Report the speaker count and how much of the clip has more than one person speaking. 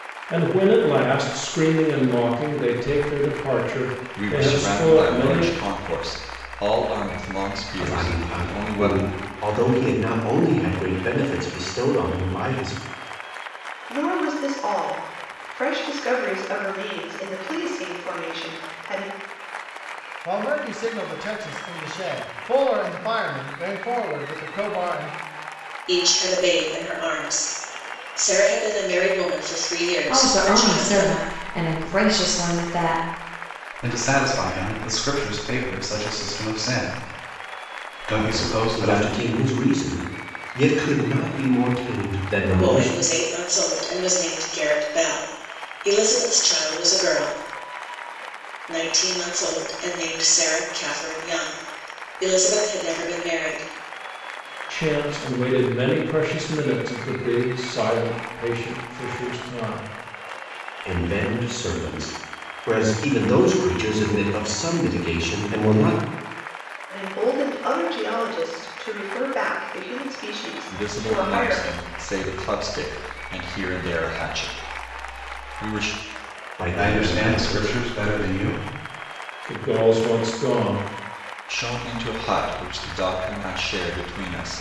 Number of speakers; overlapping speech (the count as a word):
eight, about 9%